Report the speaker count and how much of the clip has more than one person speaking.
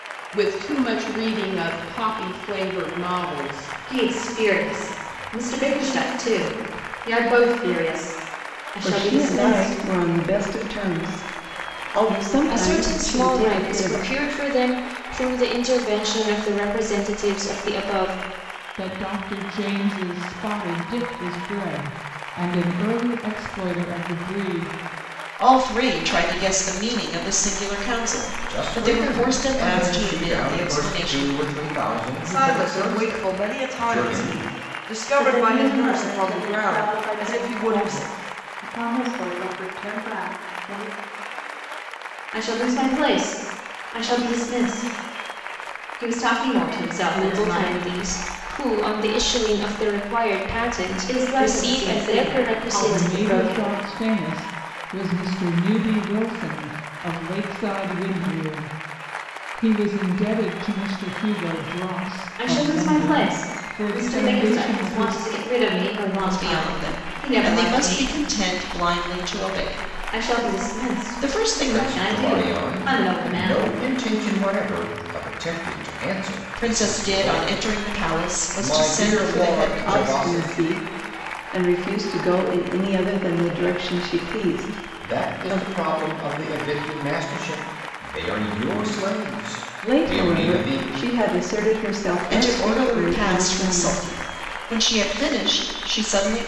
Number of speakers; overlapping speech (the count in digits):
9, about 32%